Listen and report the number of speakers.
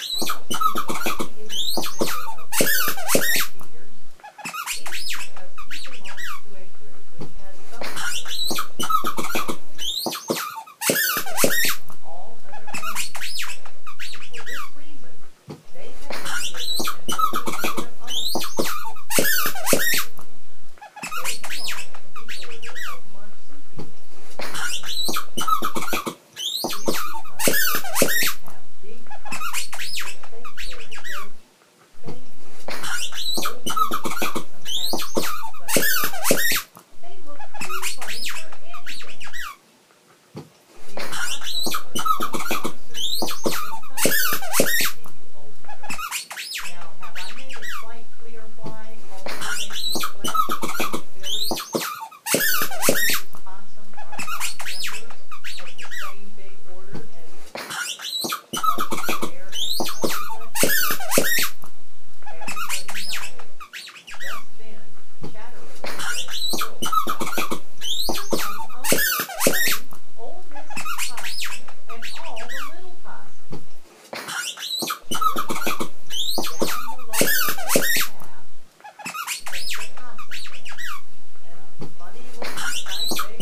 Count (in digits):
1